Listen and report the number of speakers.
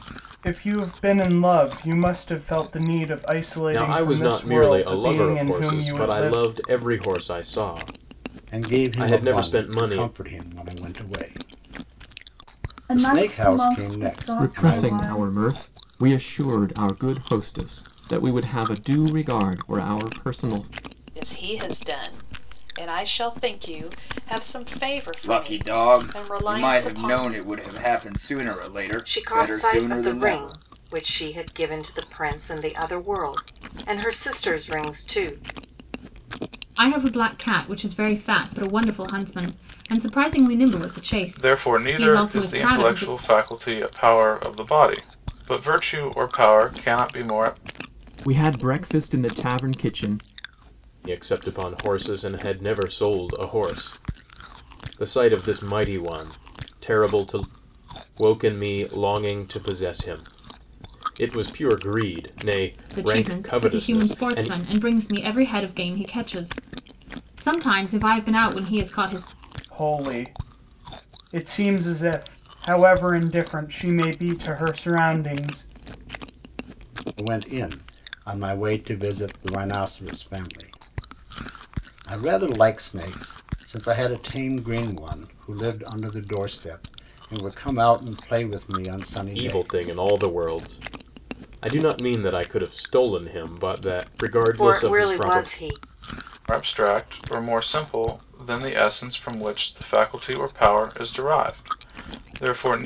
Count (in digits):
10